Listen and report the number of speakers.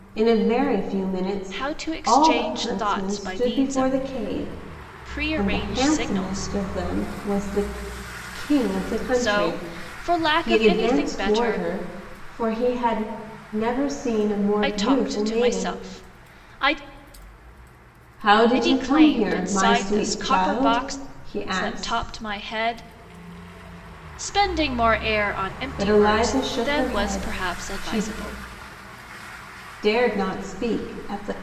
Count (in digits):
2